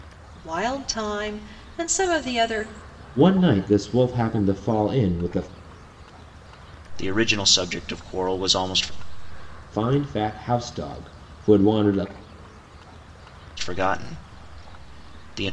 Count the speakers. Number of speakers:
3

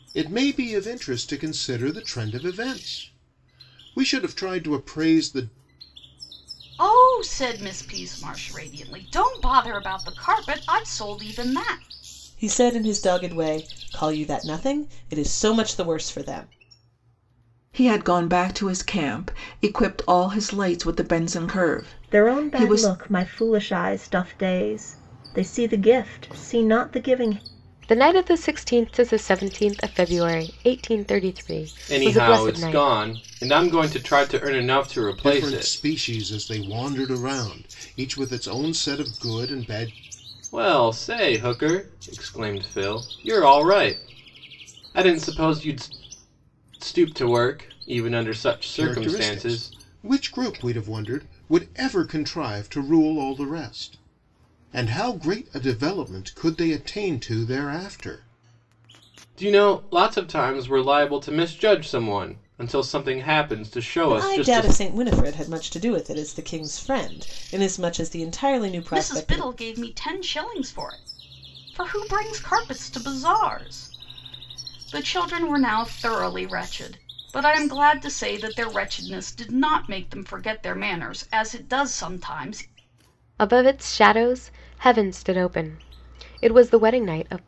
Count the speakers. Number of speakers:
7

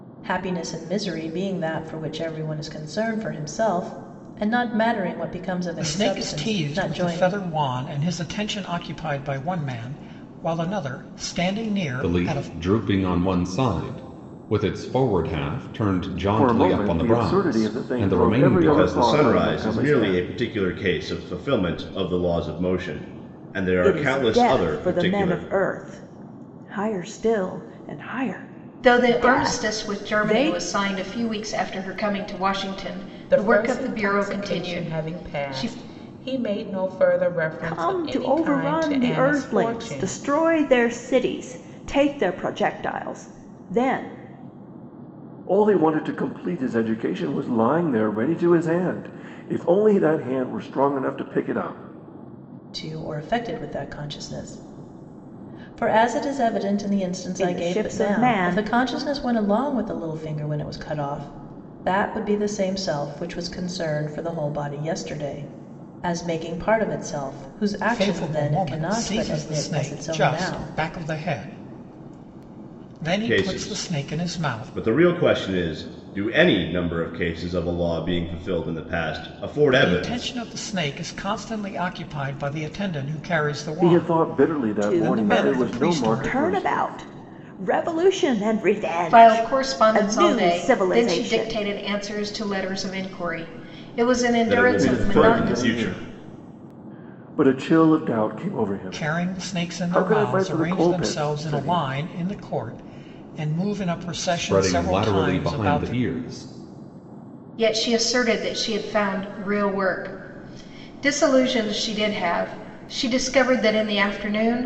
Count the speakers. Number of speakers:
8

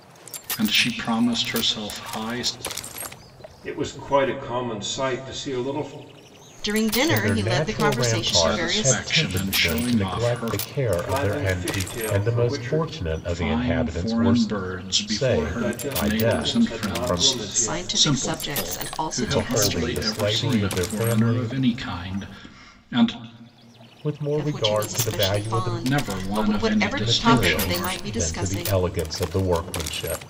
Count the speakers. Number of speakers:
4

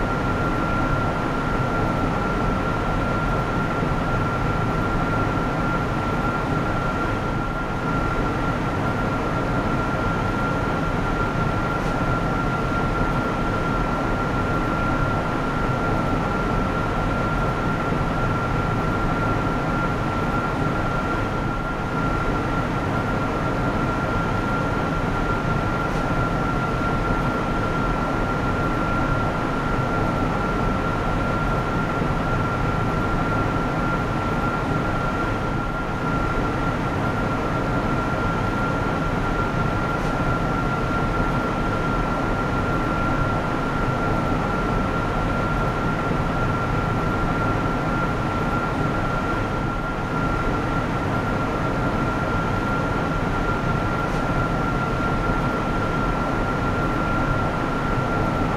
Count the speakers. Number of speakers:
0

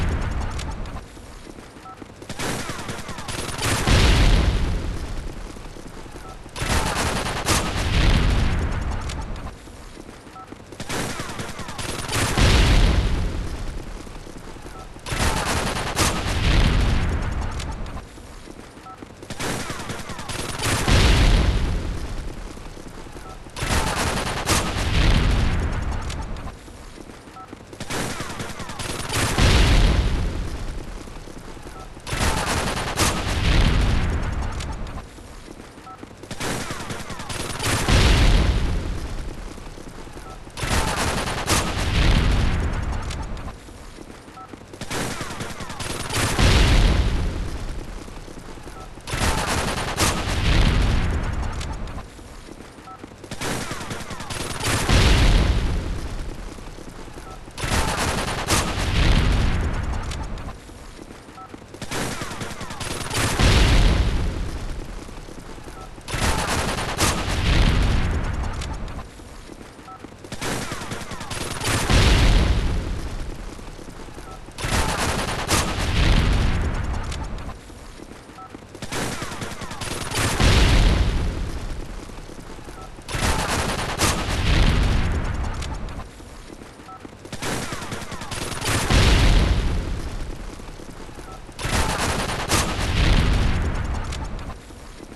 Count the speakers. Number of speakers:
0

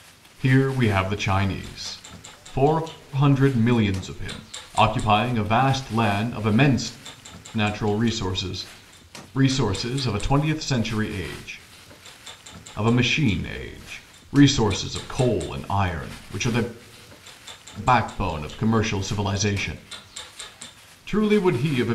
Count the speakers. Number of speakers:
1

